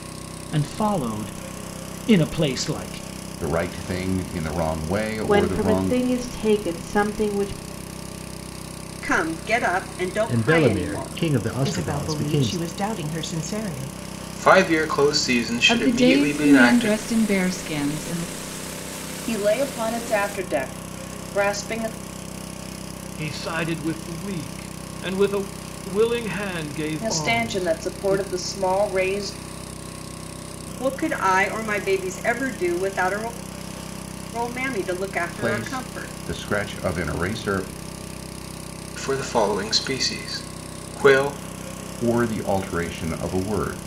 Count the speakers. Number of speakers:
ten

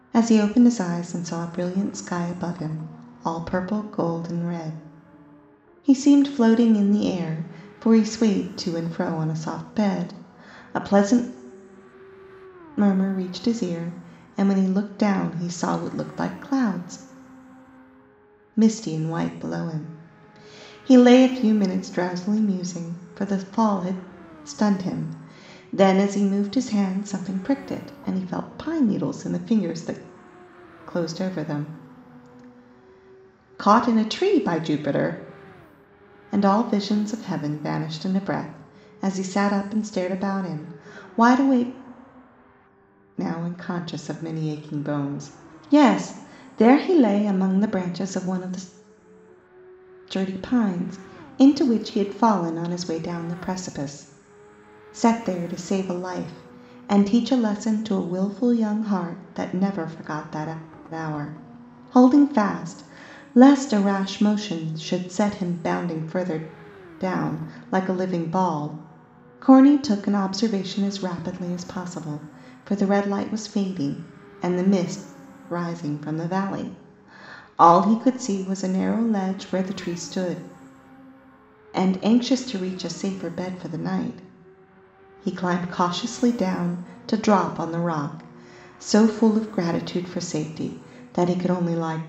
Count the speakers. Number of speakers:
one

